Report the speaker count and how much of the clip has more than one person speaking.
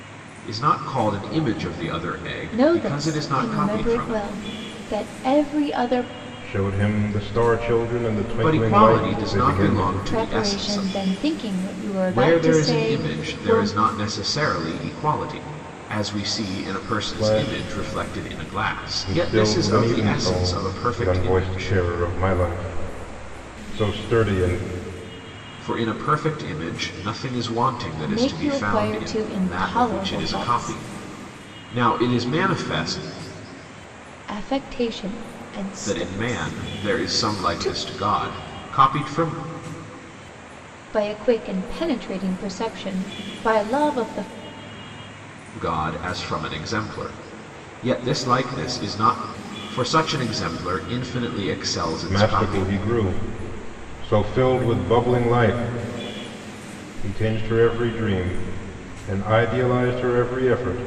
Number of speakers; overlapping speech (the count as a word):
three, about 27%